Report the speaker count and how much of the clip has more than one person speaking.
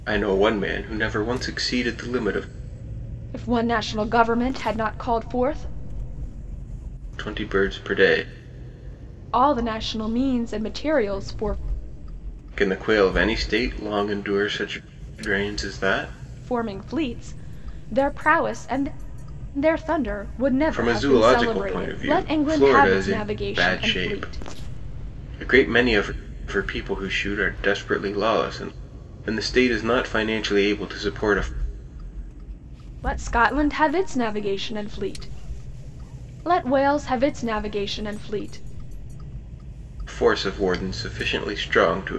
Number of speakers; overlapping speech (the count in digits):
2, about 8%